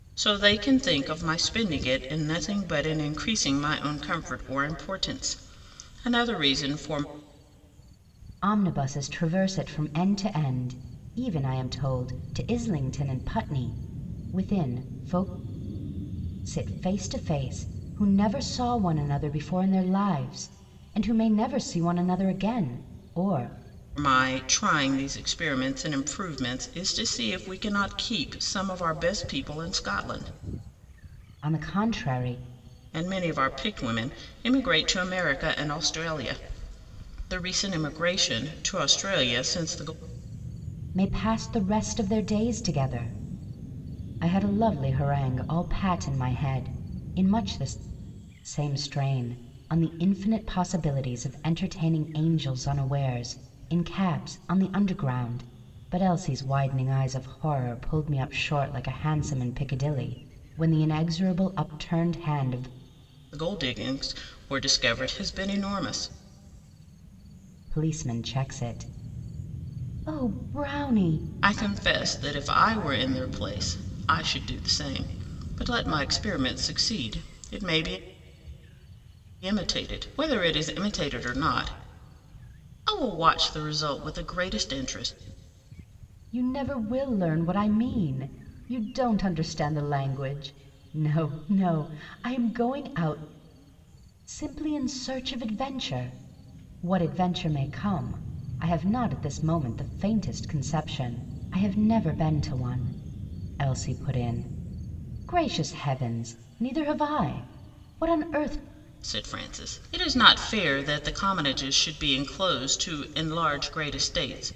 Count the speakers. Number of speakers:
2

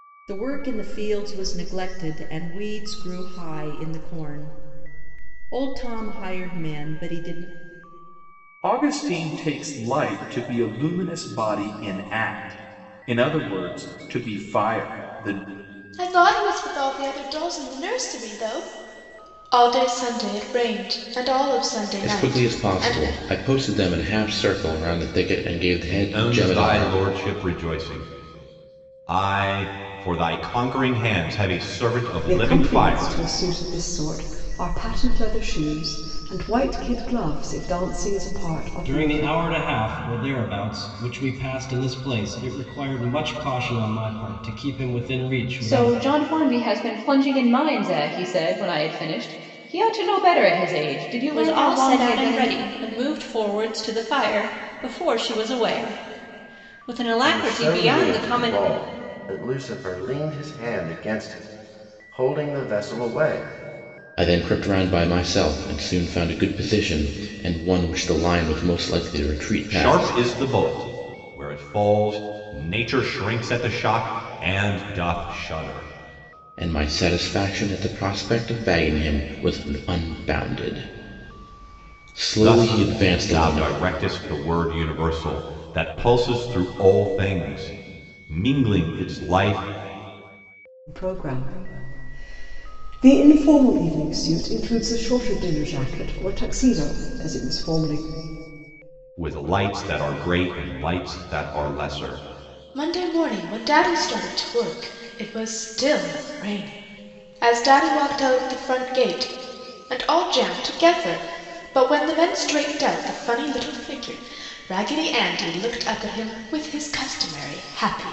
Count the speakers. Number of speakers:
10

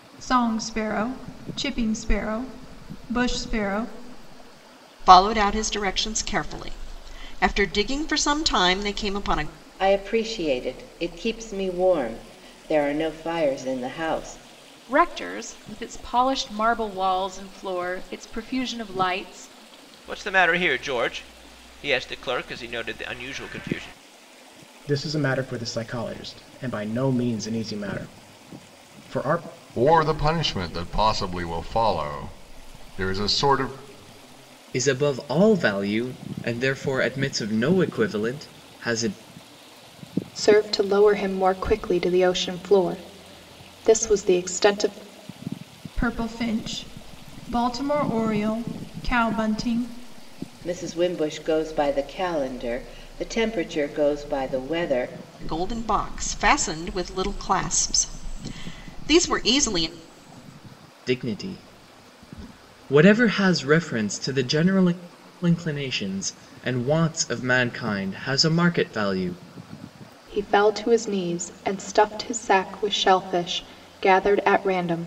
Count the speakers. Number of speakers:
9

